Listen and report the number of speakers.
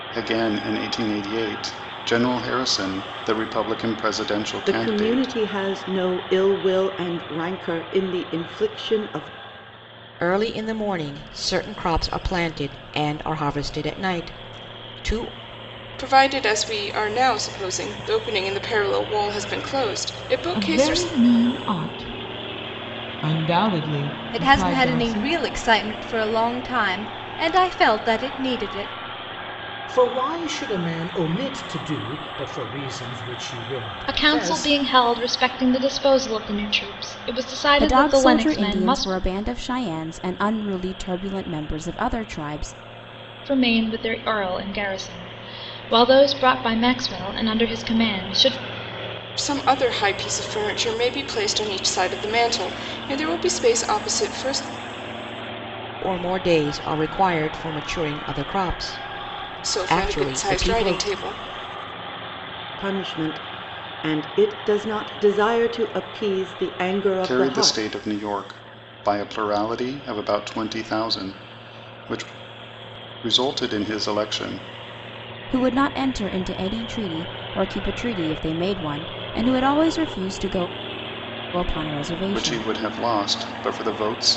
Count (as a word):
nine